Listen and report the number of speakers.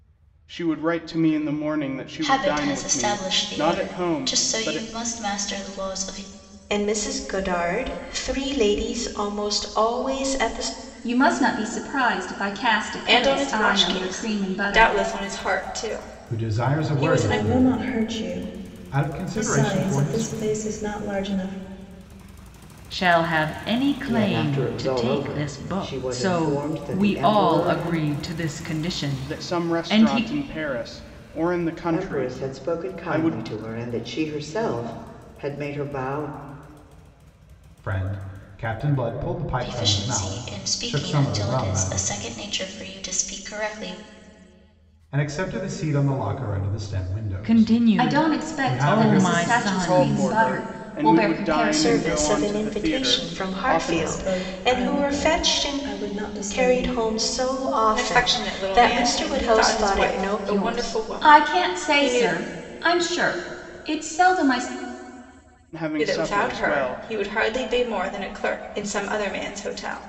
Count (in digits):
9